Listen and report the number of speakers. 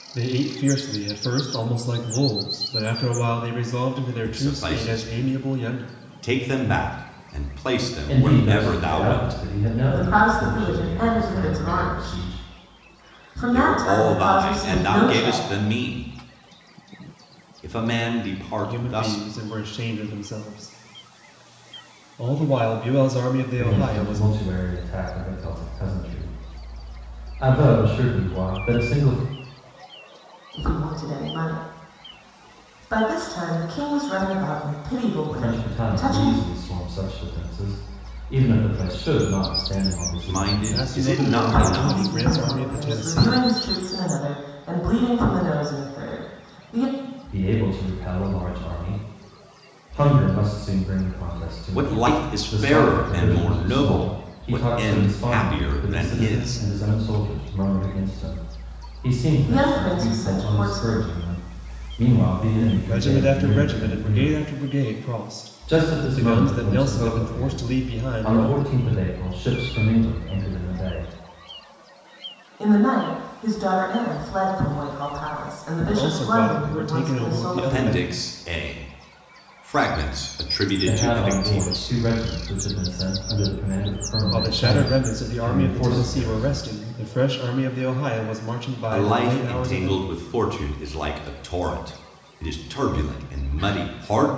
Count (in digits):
4